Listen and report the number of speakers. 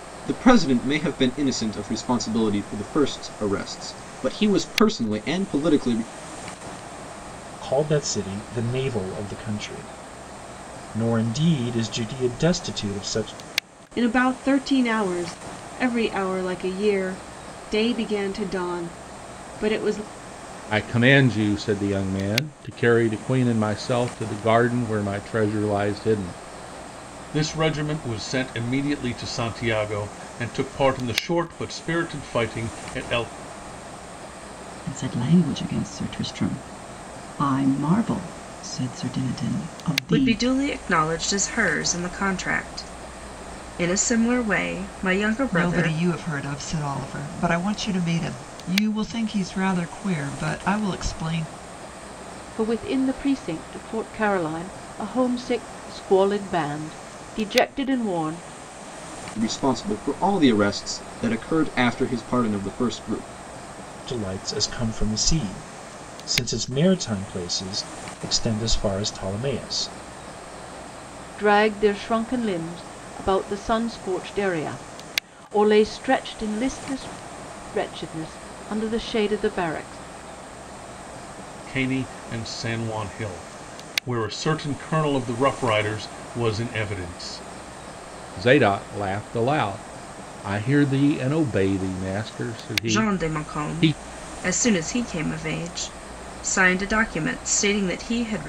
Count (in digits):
9